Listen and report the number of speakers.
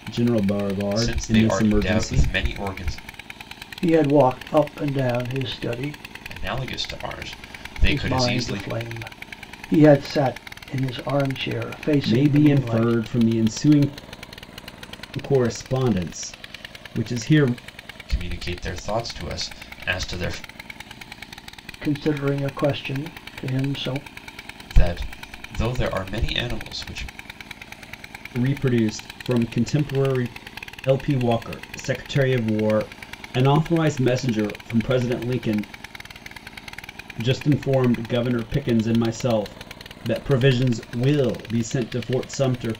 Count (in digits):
3